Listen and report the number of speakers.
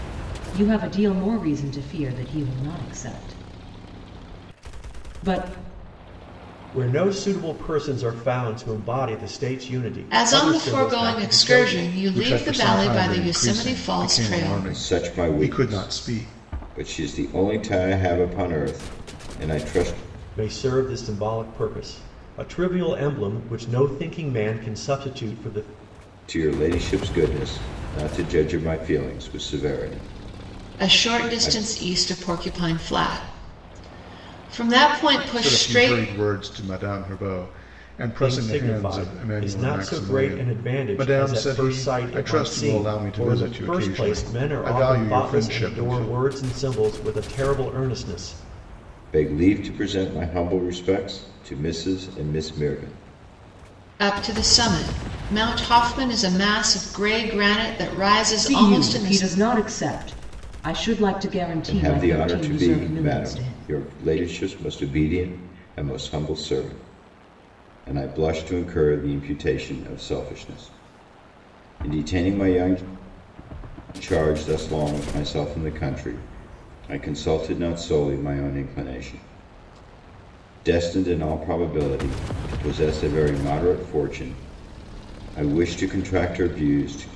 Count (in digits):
5